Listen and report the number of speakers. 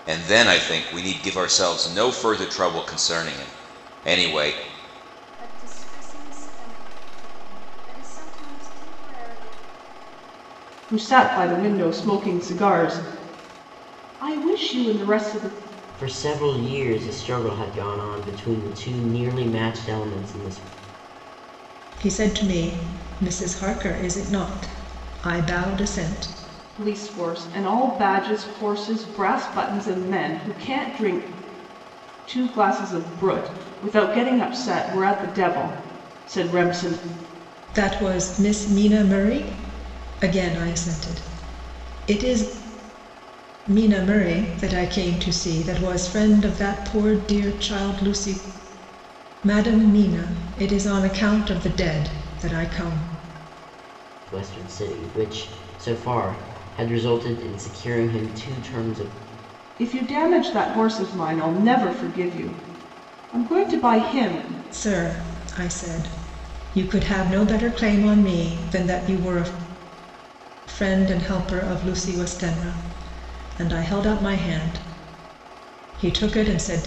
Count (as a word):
five